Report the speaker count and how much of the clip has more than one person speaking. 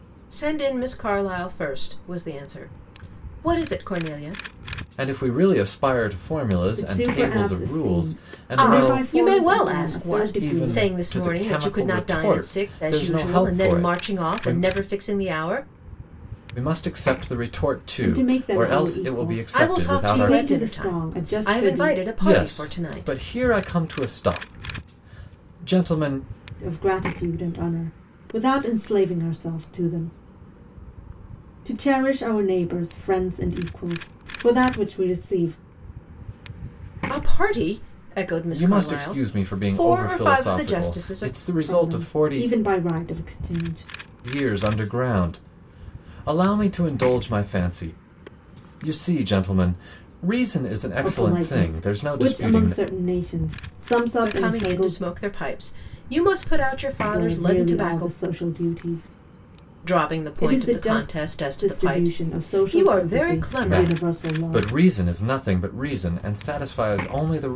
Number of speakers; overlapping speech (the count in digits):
3, about 37%